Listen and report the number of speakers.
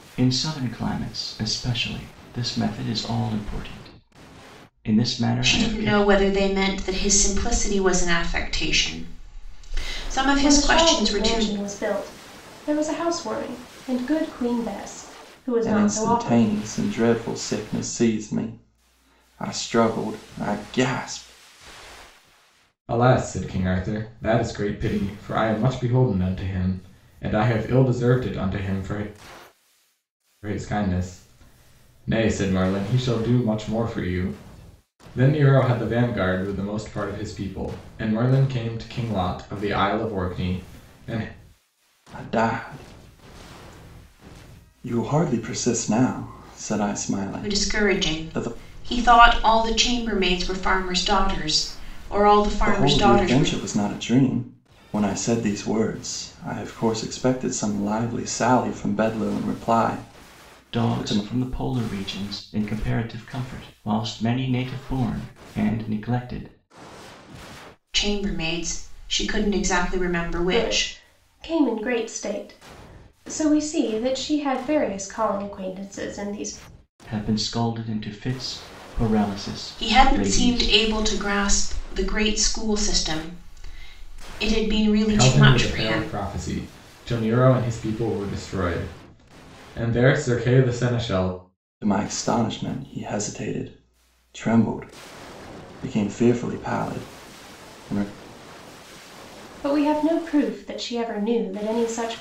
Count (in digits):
5